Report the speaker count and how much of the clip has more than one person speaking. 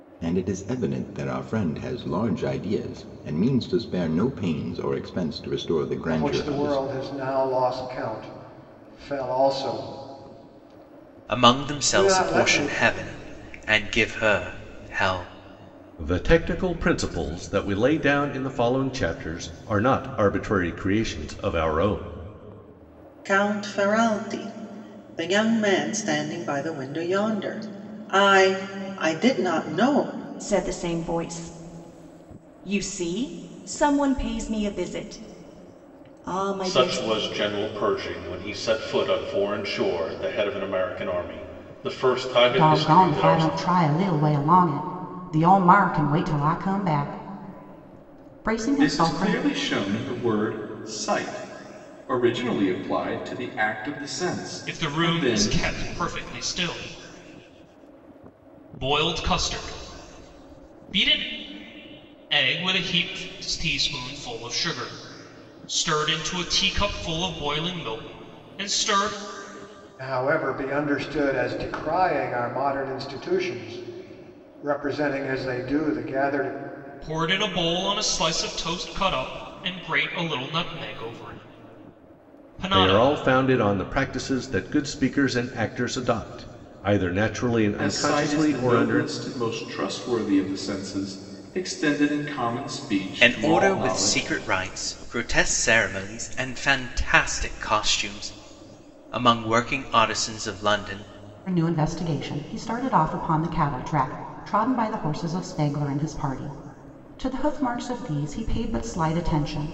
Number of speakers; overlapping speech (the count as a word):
ten, about 7%